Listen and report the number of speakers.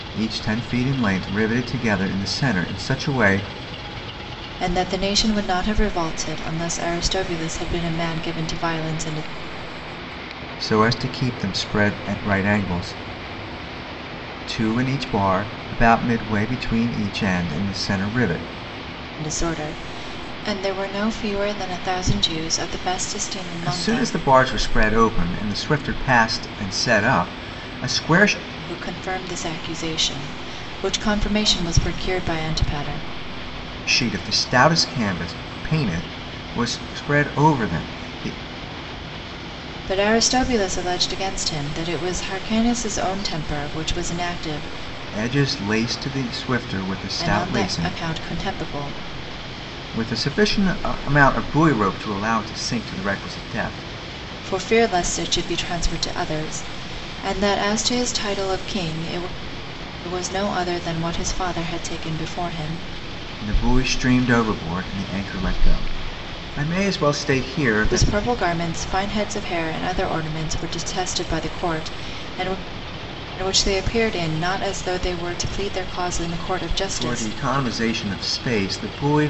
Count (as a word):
two